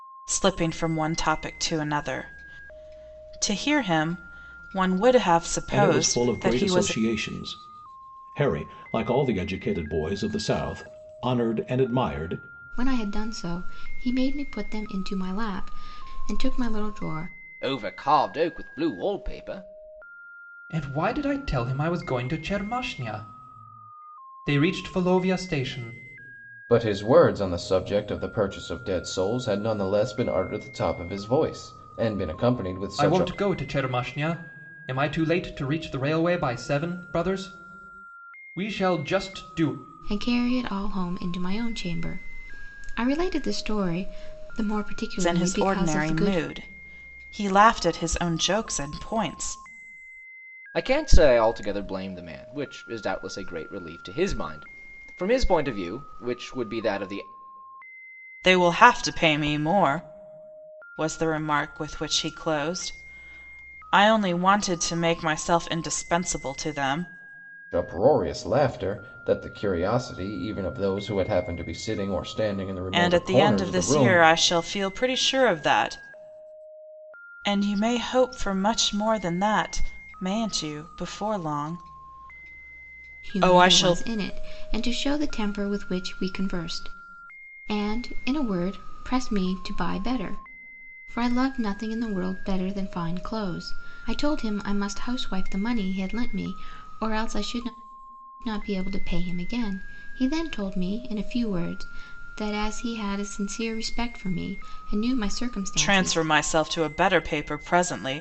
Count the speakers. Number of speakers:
six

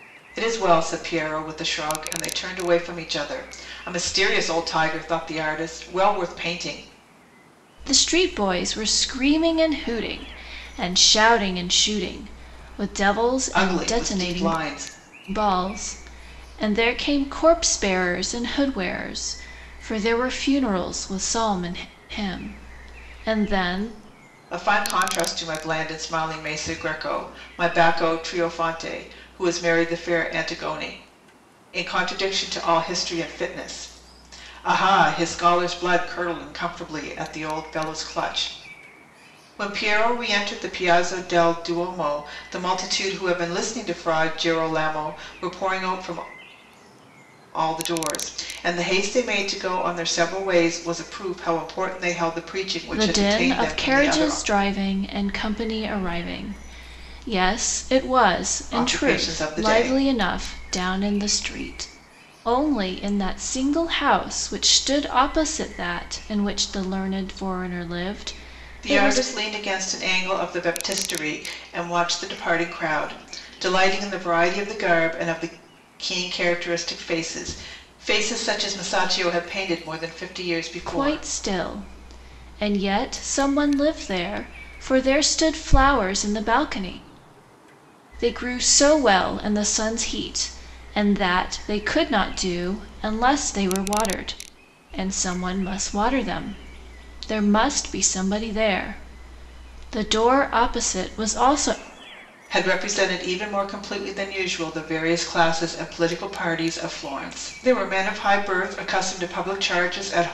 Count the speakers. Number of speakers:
two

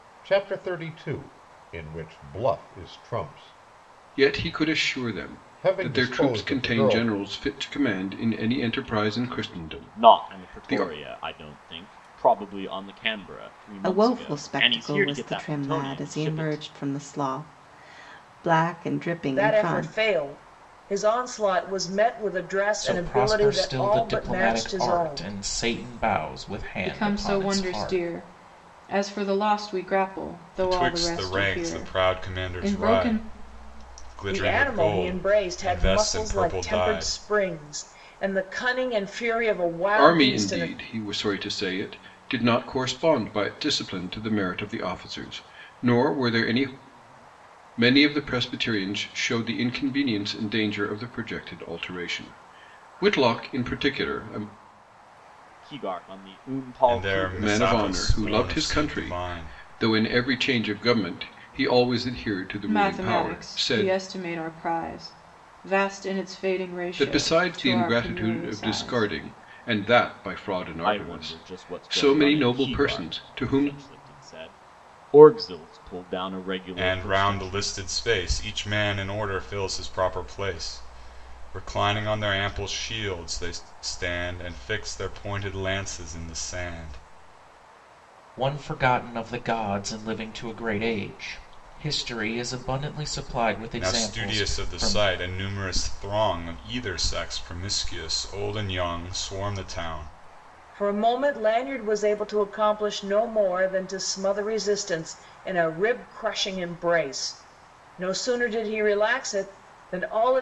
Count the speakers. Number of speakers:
eight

